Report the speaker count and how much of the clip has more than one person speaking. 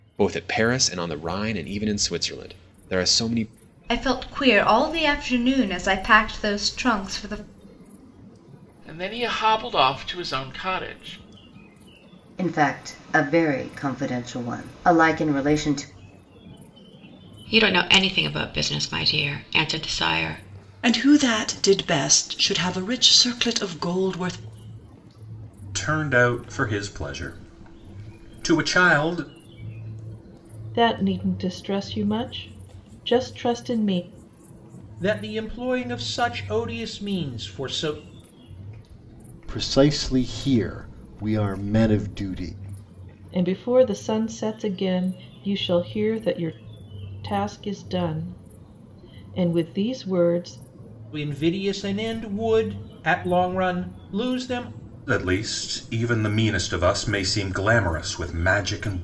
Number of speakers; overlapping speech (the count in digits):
10, no overlap